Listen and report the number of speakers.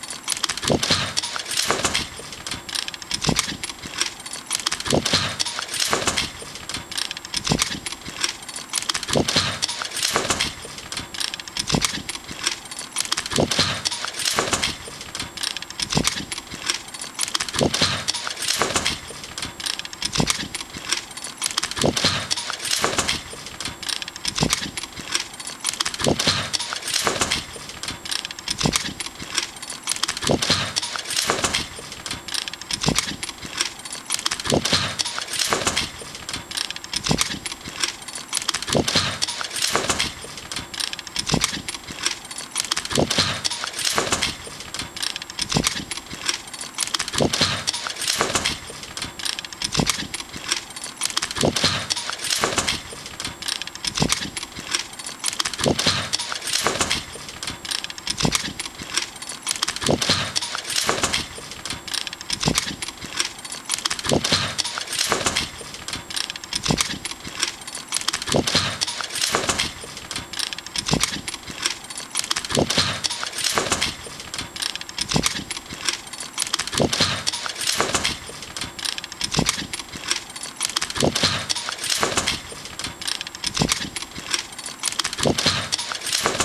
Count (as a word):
zero